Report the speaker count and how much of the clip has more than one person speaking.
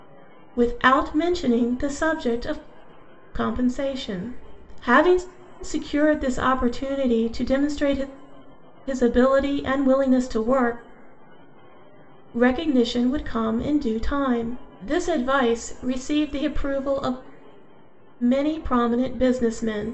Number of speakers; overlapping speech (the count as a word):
one, no overlap